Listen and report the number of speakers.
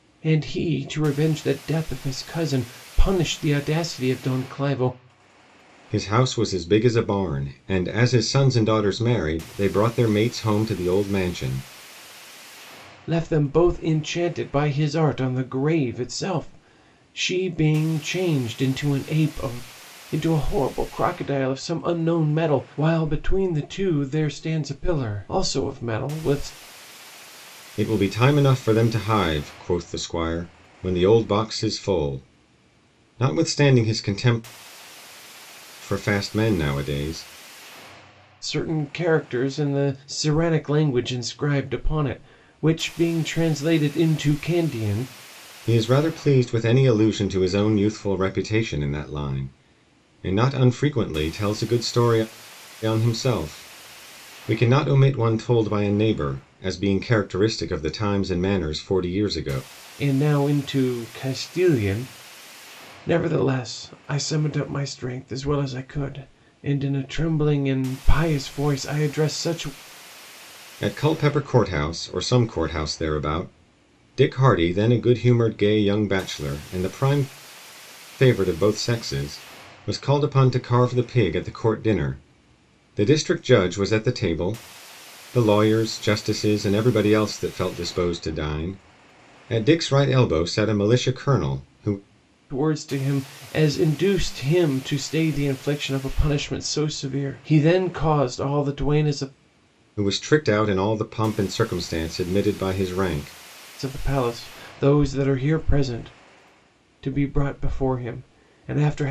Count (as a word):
two